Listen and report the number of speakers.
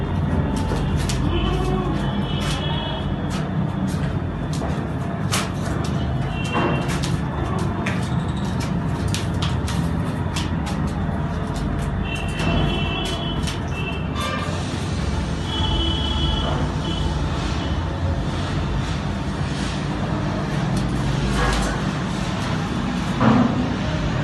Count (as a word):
zero